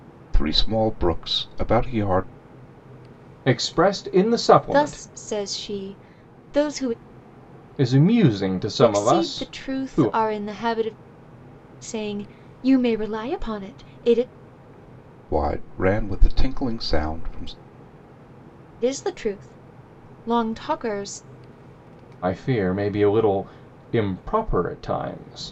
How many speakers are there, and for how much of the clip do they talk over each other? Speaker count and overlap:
three, about 7%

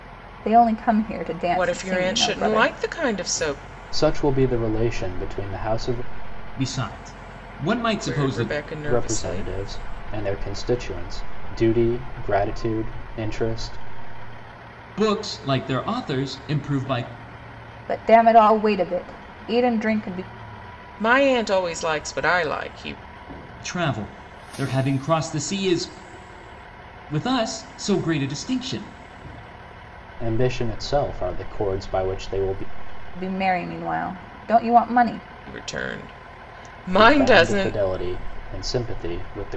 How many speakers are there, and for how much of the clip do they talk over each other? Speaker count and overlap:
four, about 9%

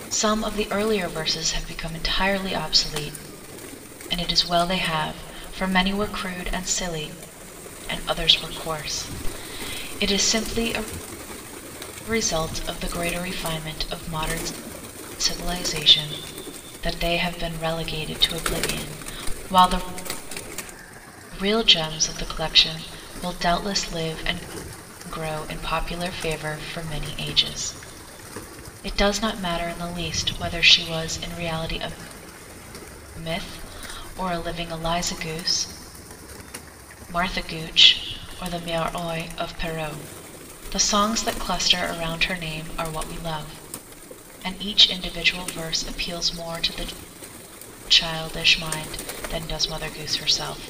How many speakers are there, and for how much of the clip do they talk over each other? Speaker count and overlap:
one, no overlap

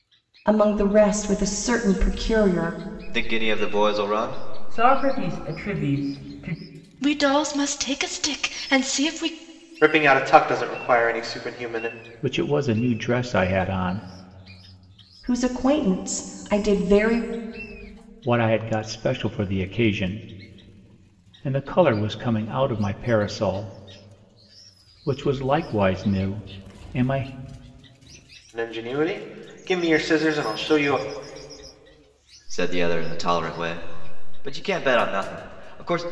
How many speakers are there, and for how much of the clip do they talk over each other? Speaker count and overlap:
six, no overlap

